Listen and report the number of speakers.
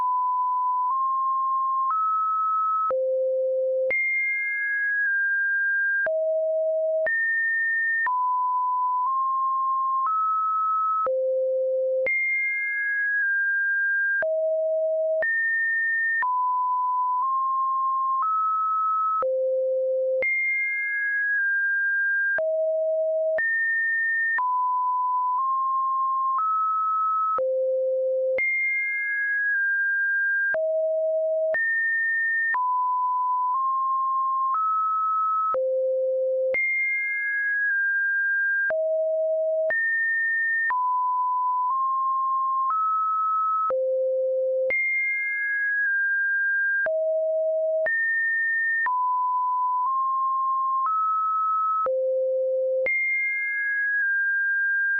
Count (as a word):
zero